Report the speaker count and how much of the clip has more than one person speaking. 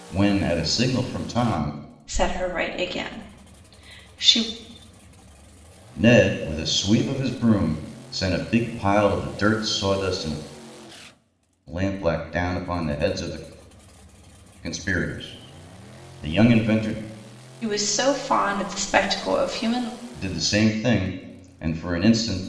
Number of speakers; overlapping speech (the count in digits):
2, no overlap